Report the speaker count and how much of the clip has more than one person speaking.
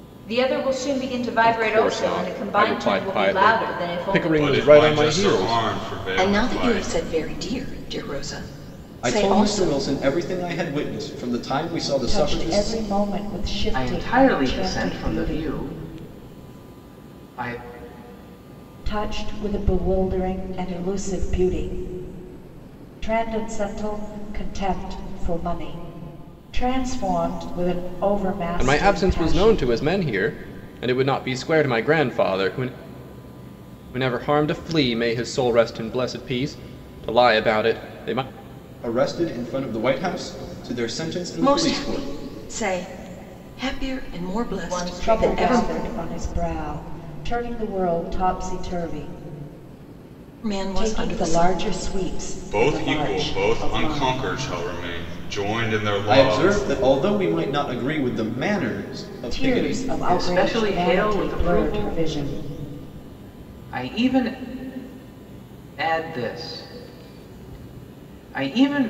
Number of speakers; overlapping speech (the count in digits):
7, about 26%